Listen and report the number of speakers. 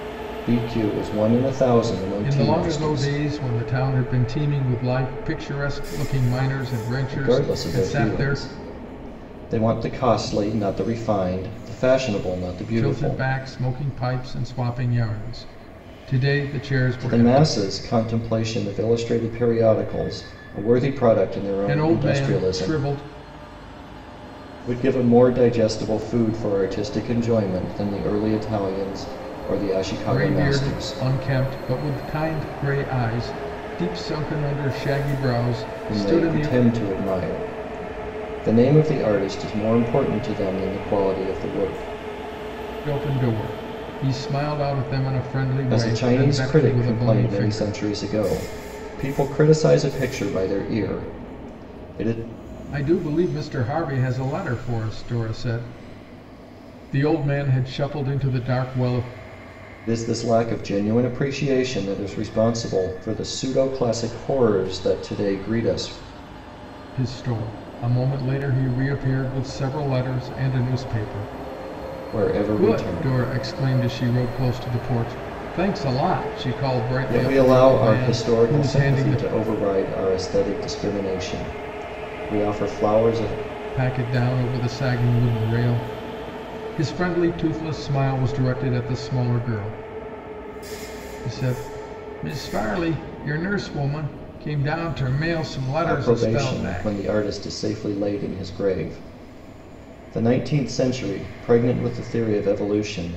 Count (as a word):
two